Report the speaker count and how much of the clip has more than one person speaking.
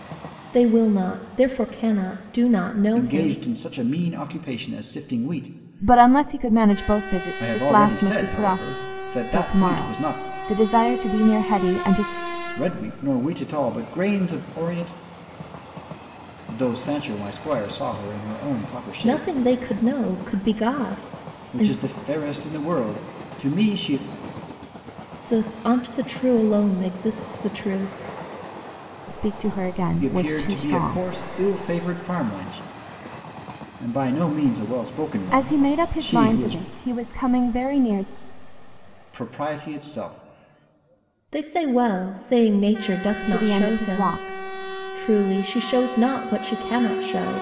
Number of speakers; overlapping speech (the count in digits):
3, about 14%